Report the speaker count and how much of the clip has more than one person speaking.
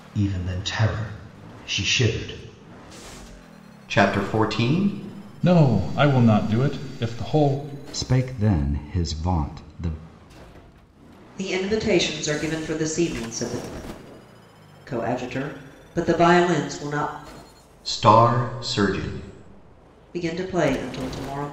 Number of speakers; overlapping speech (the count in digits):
5, no overlap